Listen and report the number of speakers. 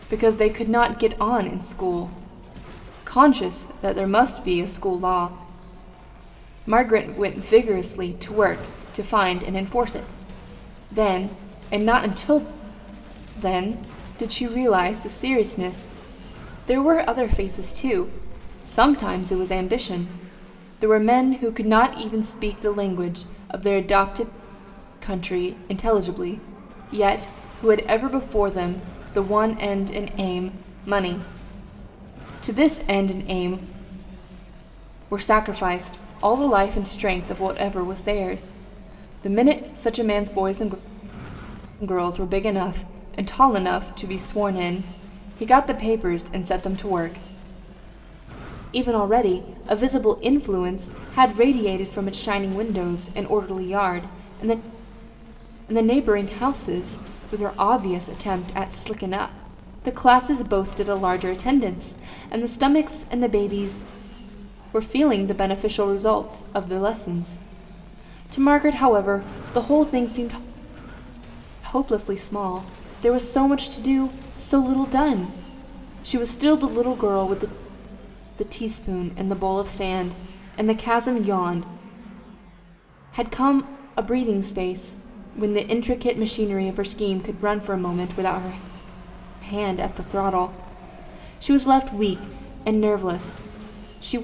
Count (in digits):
1